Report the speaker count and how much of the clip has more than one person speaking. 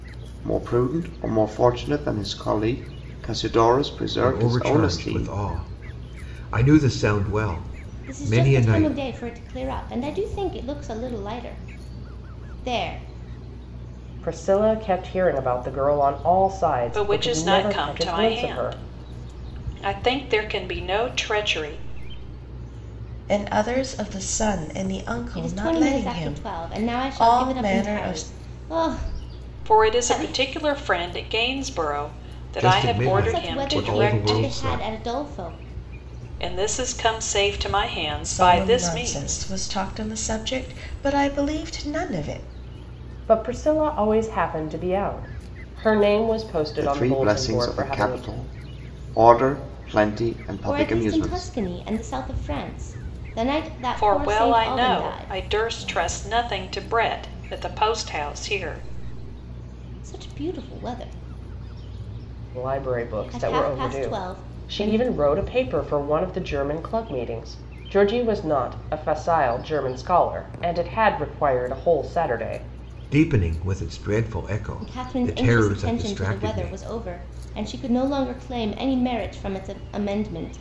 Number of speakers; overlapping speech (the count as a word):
six, about 25%